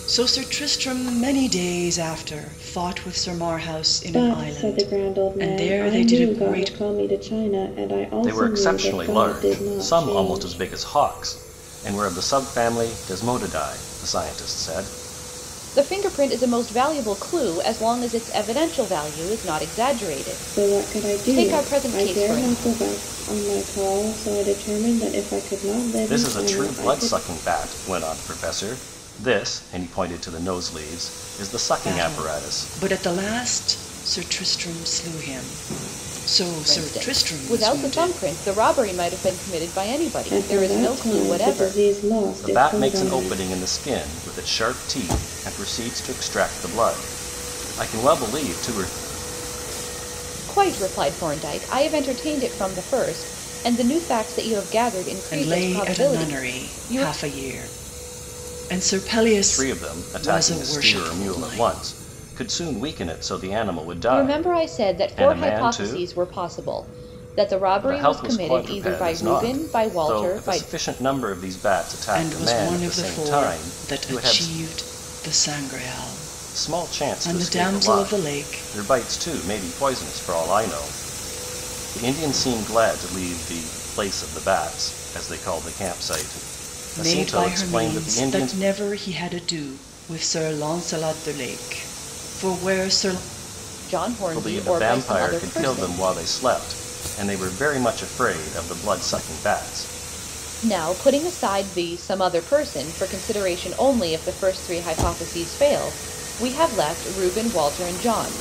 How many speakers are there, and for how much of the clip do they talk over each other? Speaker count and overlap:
4, about 28%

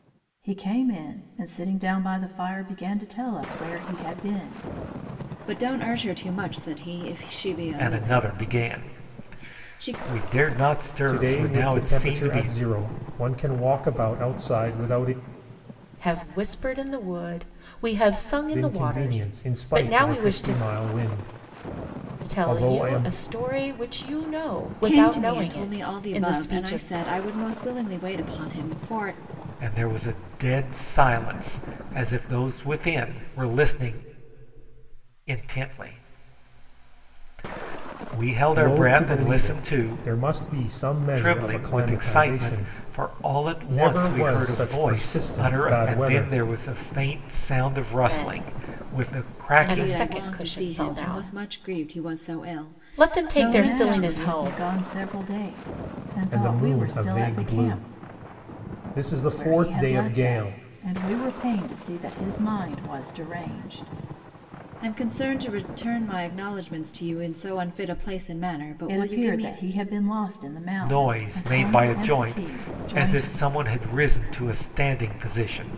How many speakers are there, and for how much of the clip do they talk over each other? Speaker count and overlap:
5, about 34%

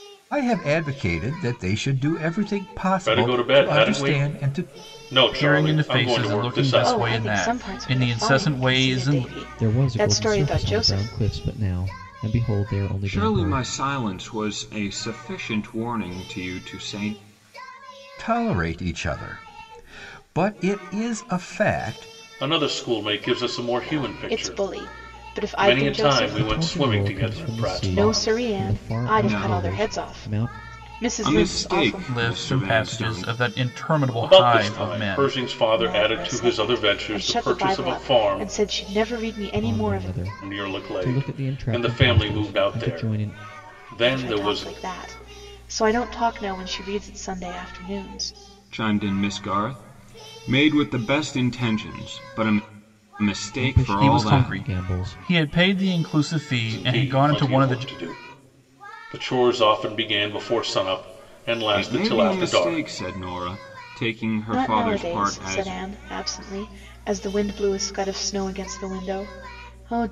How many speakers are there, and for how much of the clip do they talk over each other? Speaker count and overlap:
6, about 43%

